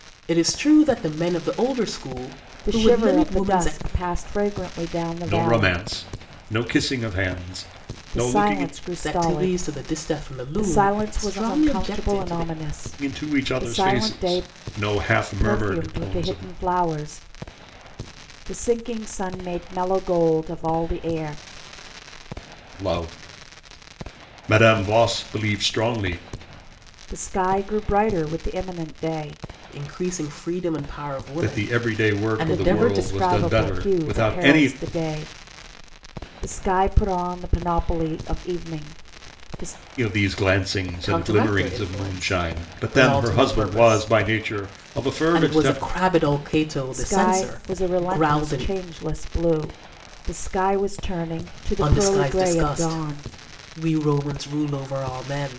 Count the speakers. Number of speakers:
3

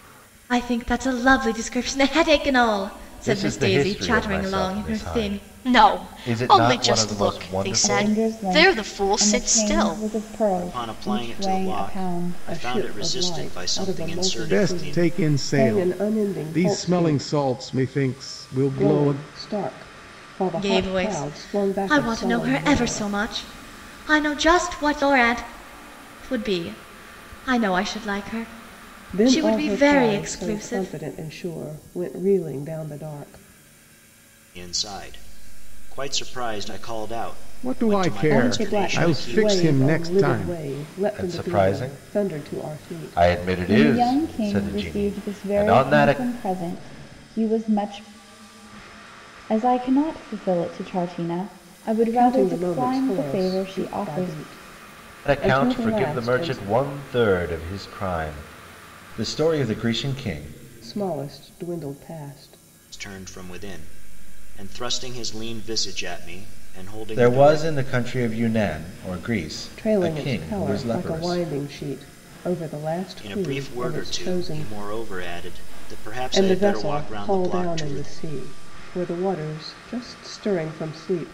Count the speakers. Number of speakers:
7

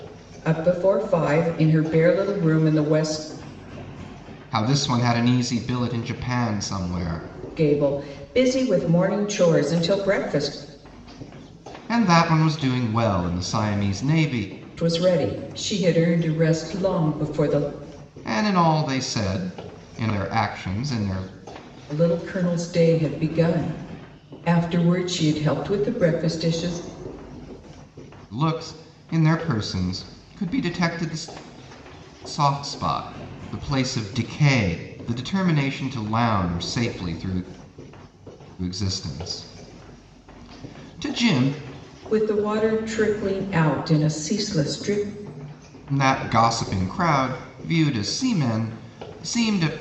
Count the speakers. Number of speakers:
2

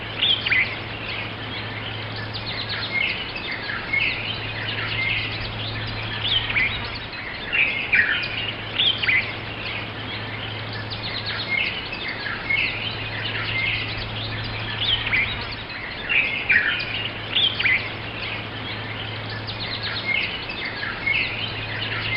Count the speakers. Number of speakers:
0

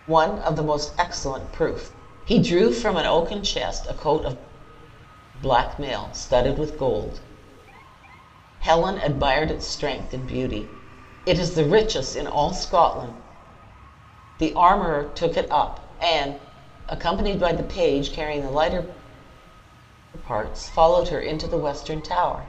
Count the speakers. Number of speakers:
1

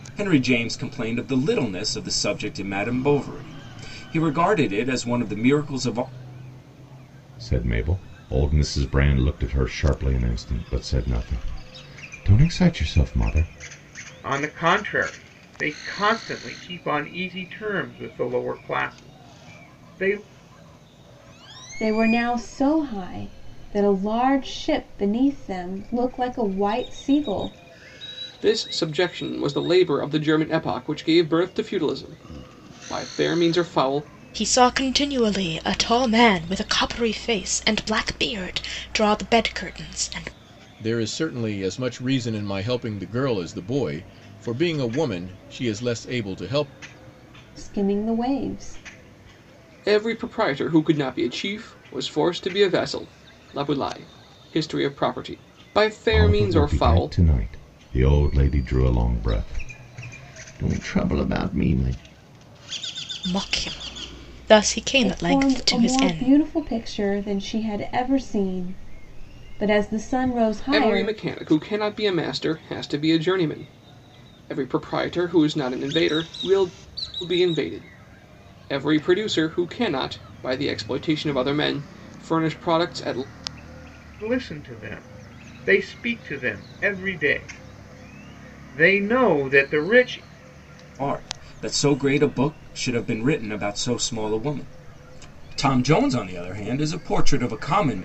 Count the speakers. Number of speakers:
7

